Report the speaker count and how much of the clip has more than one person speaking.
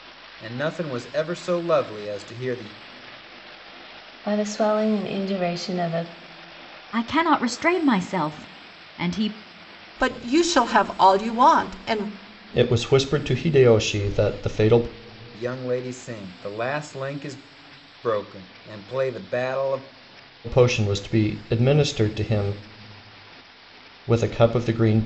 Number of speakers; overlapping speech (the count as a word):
five, no overlap